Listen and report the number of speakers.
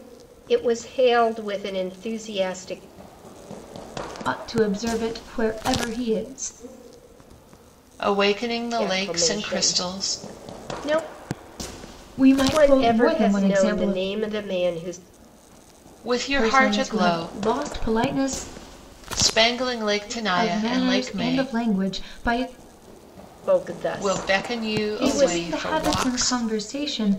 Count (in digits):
3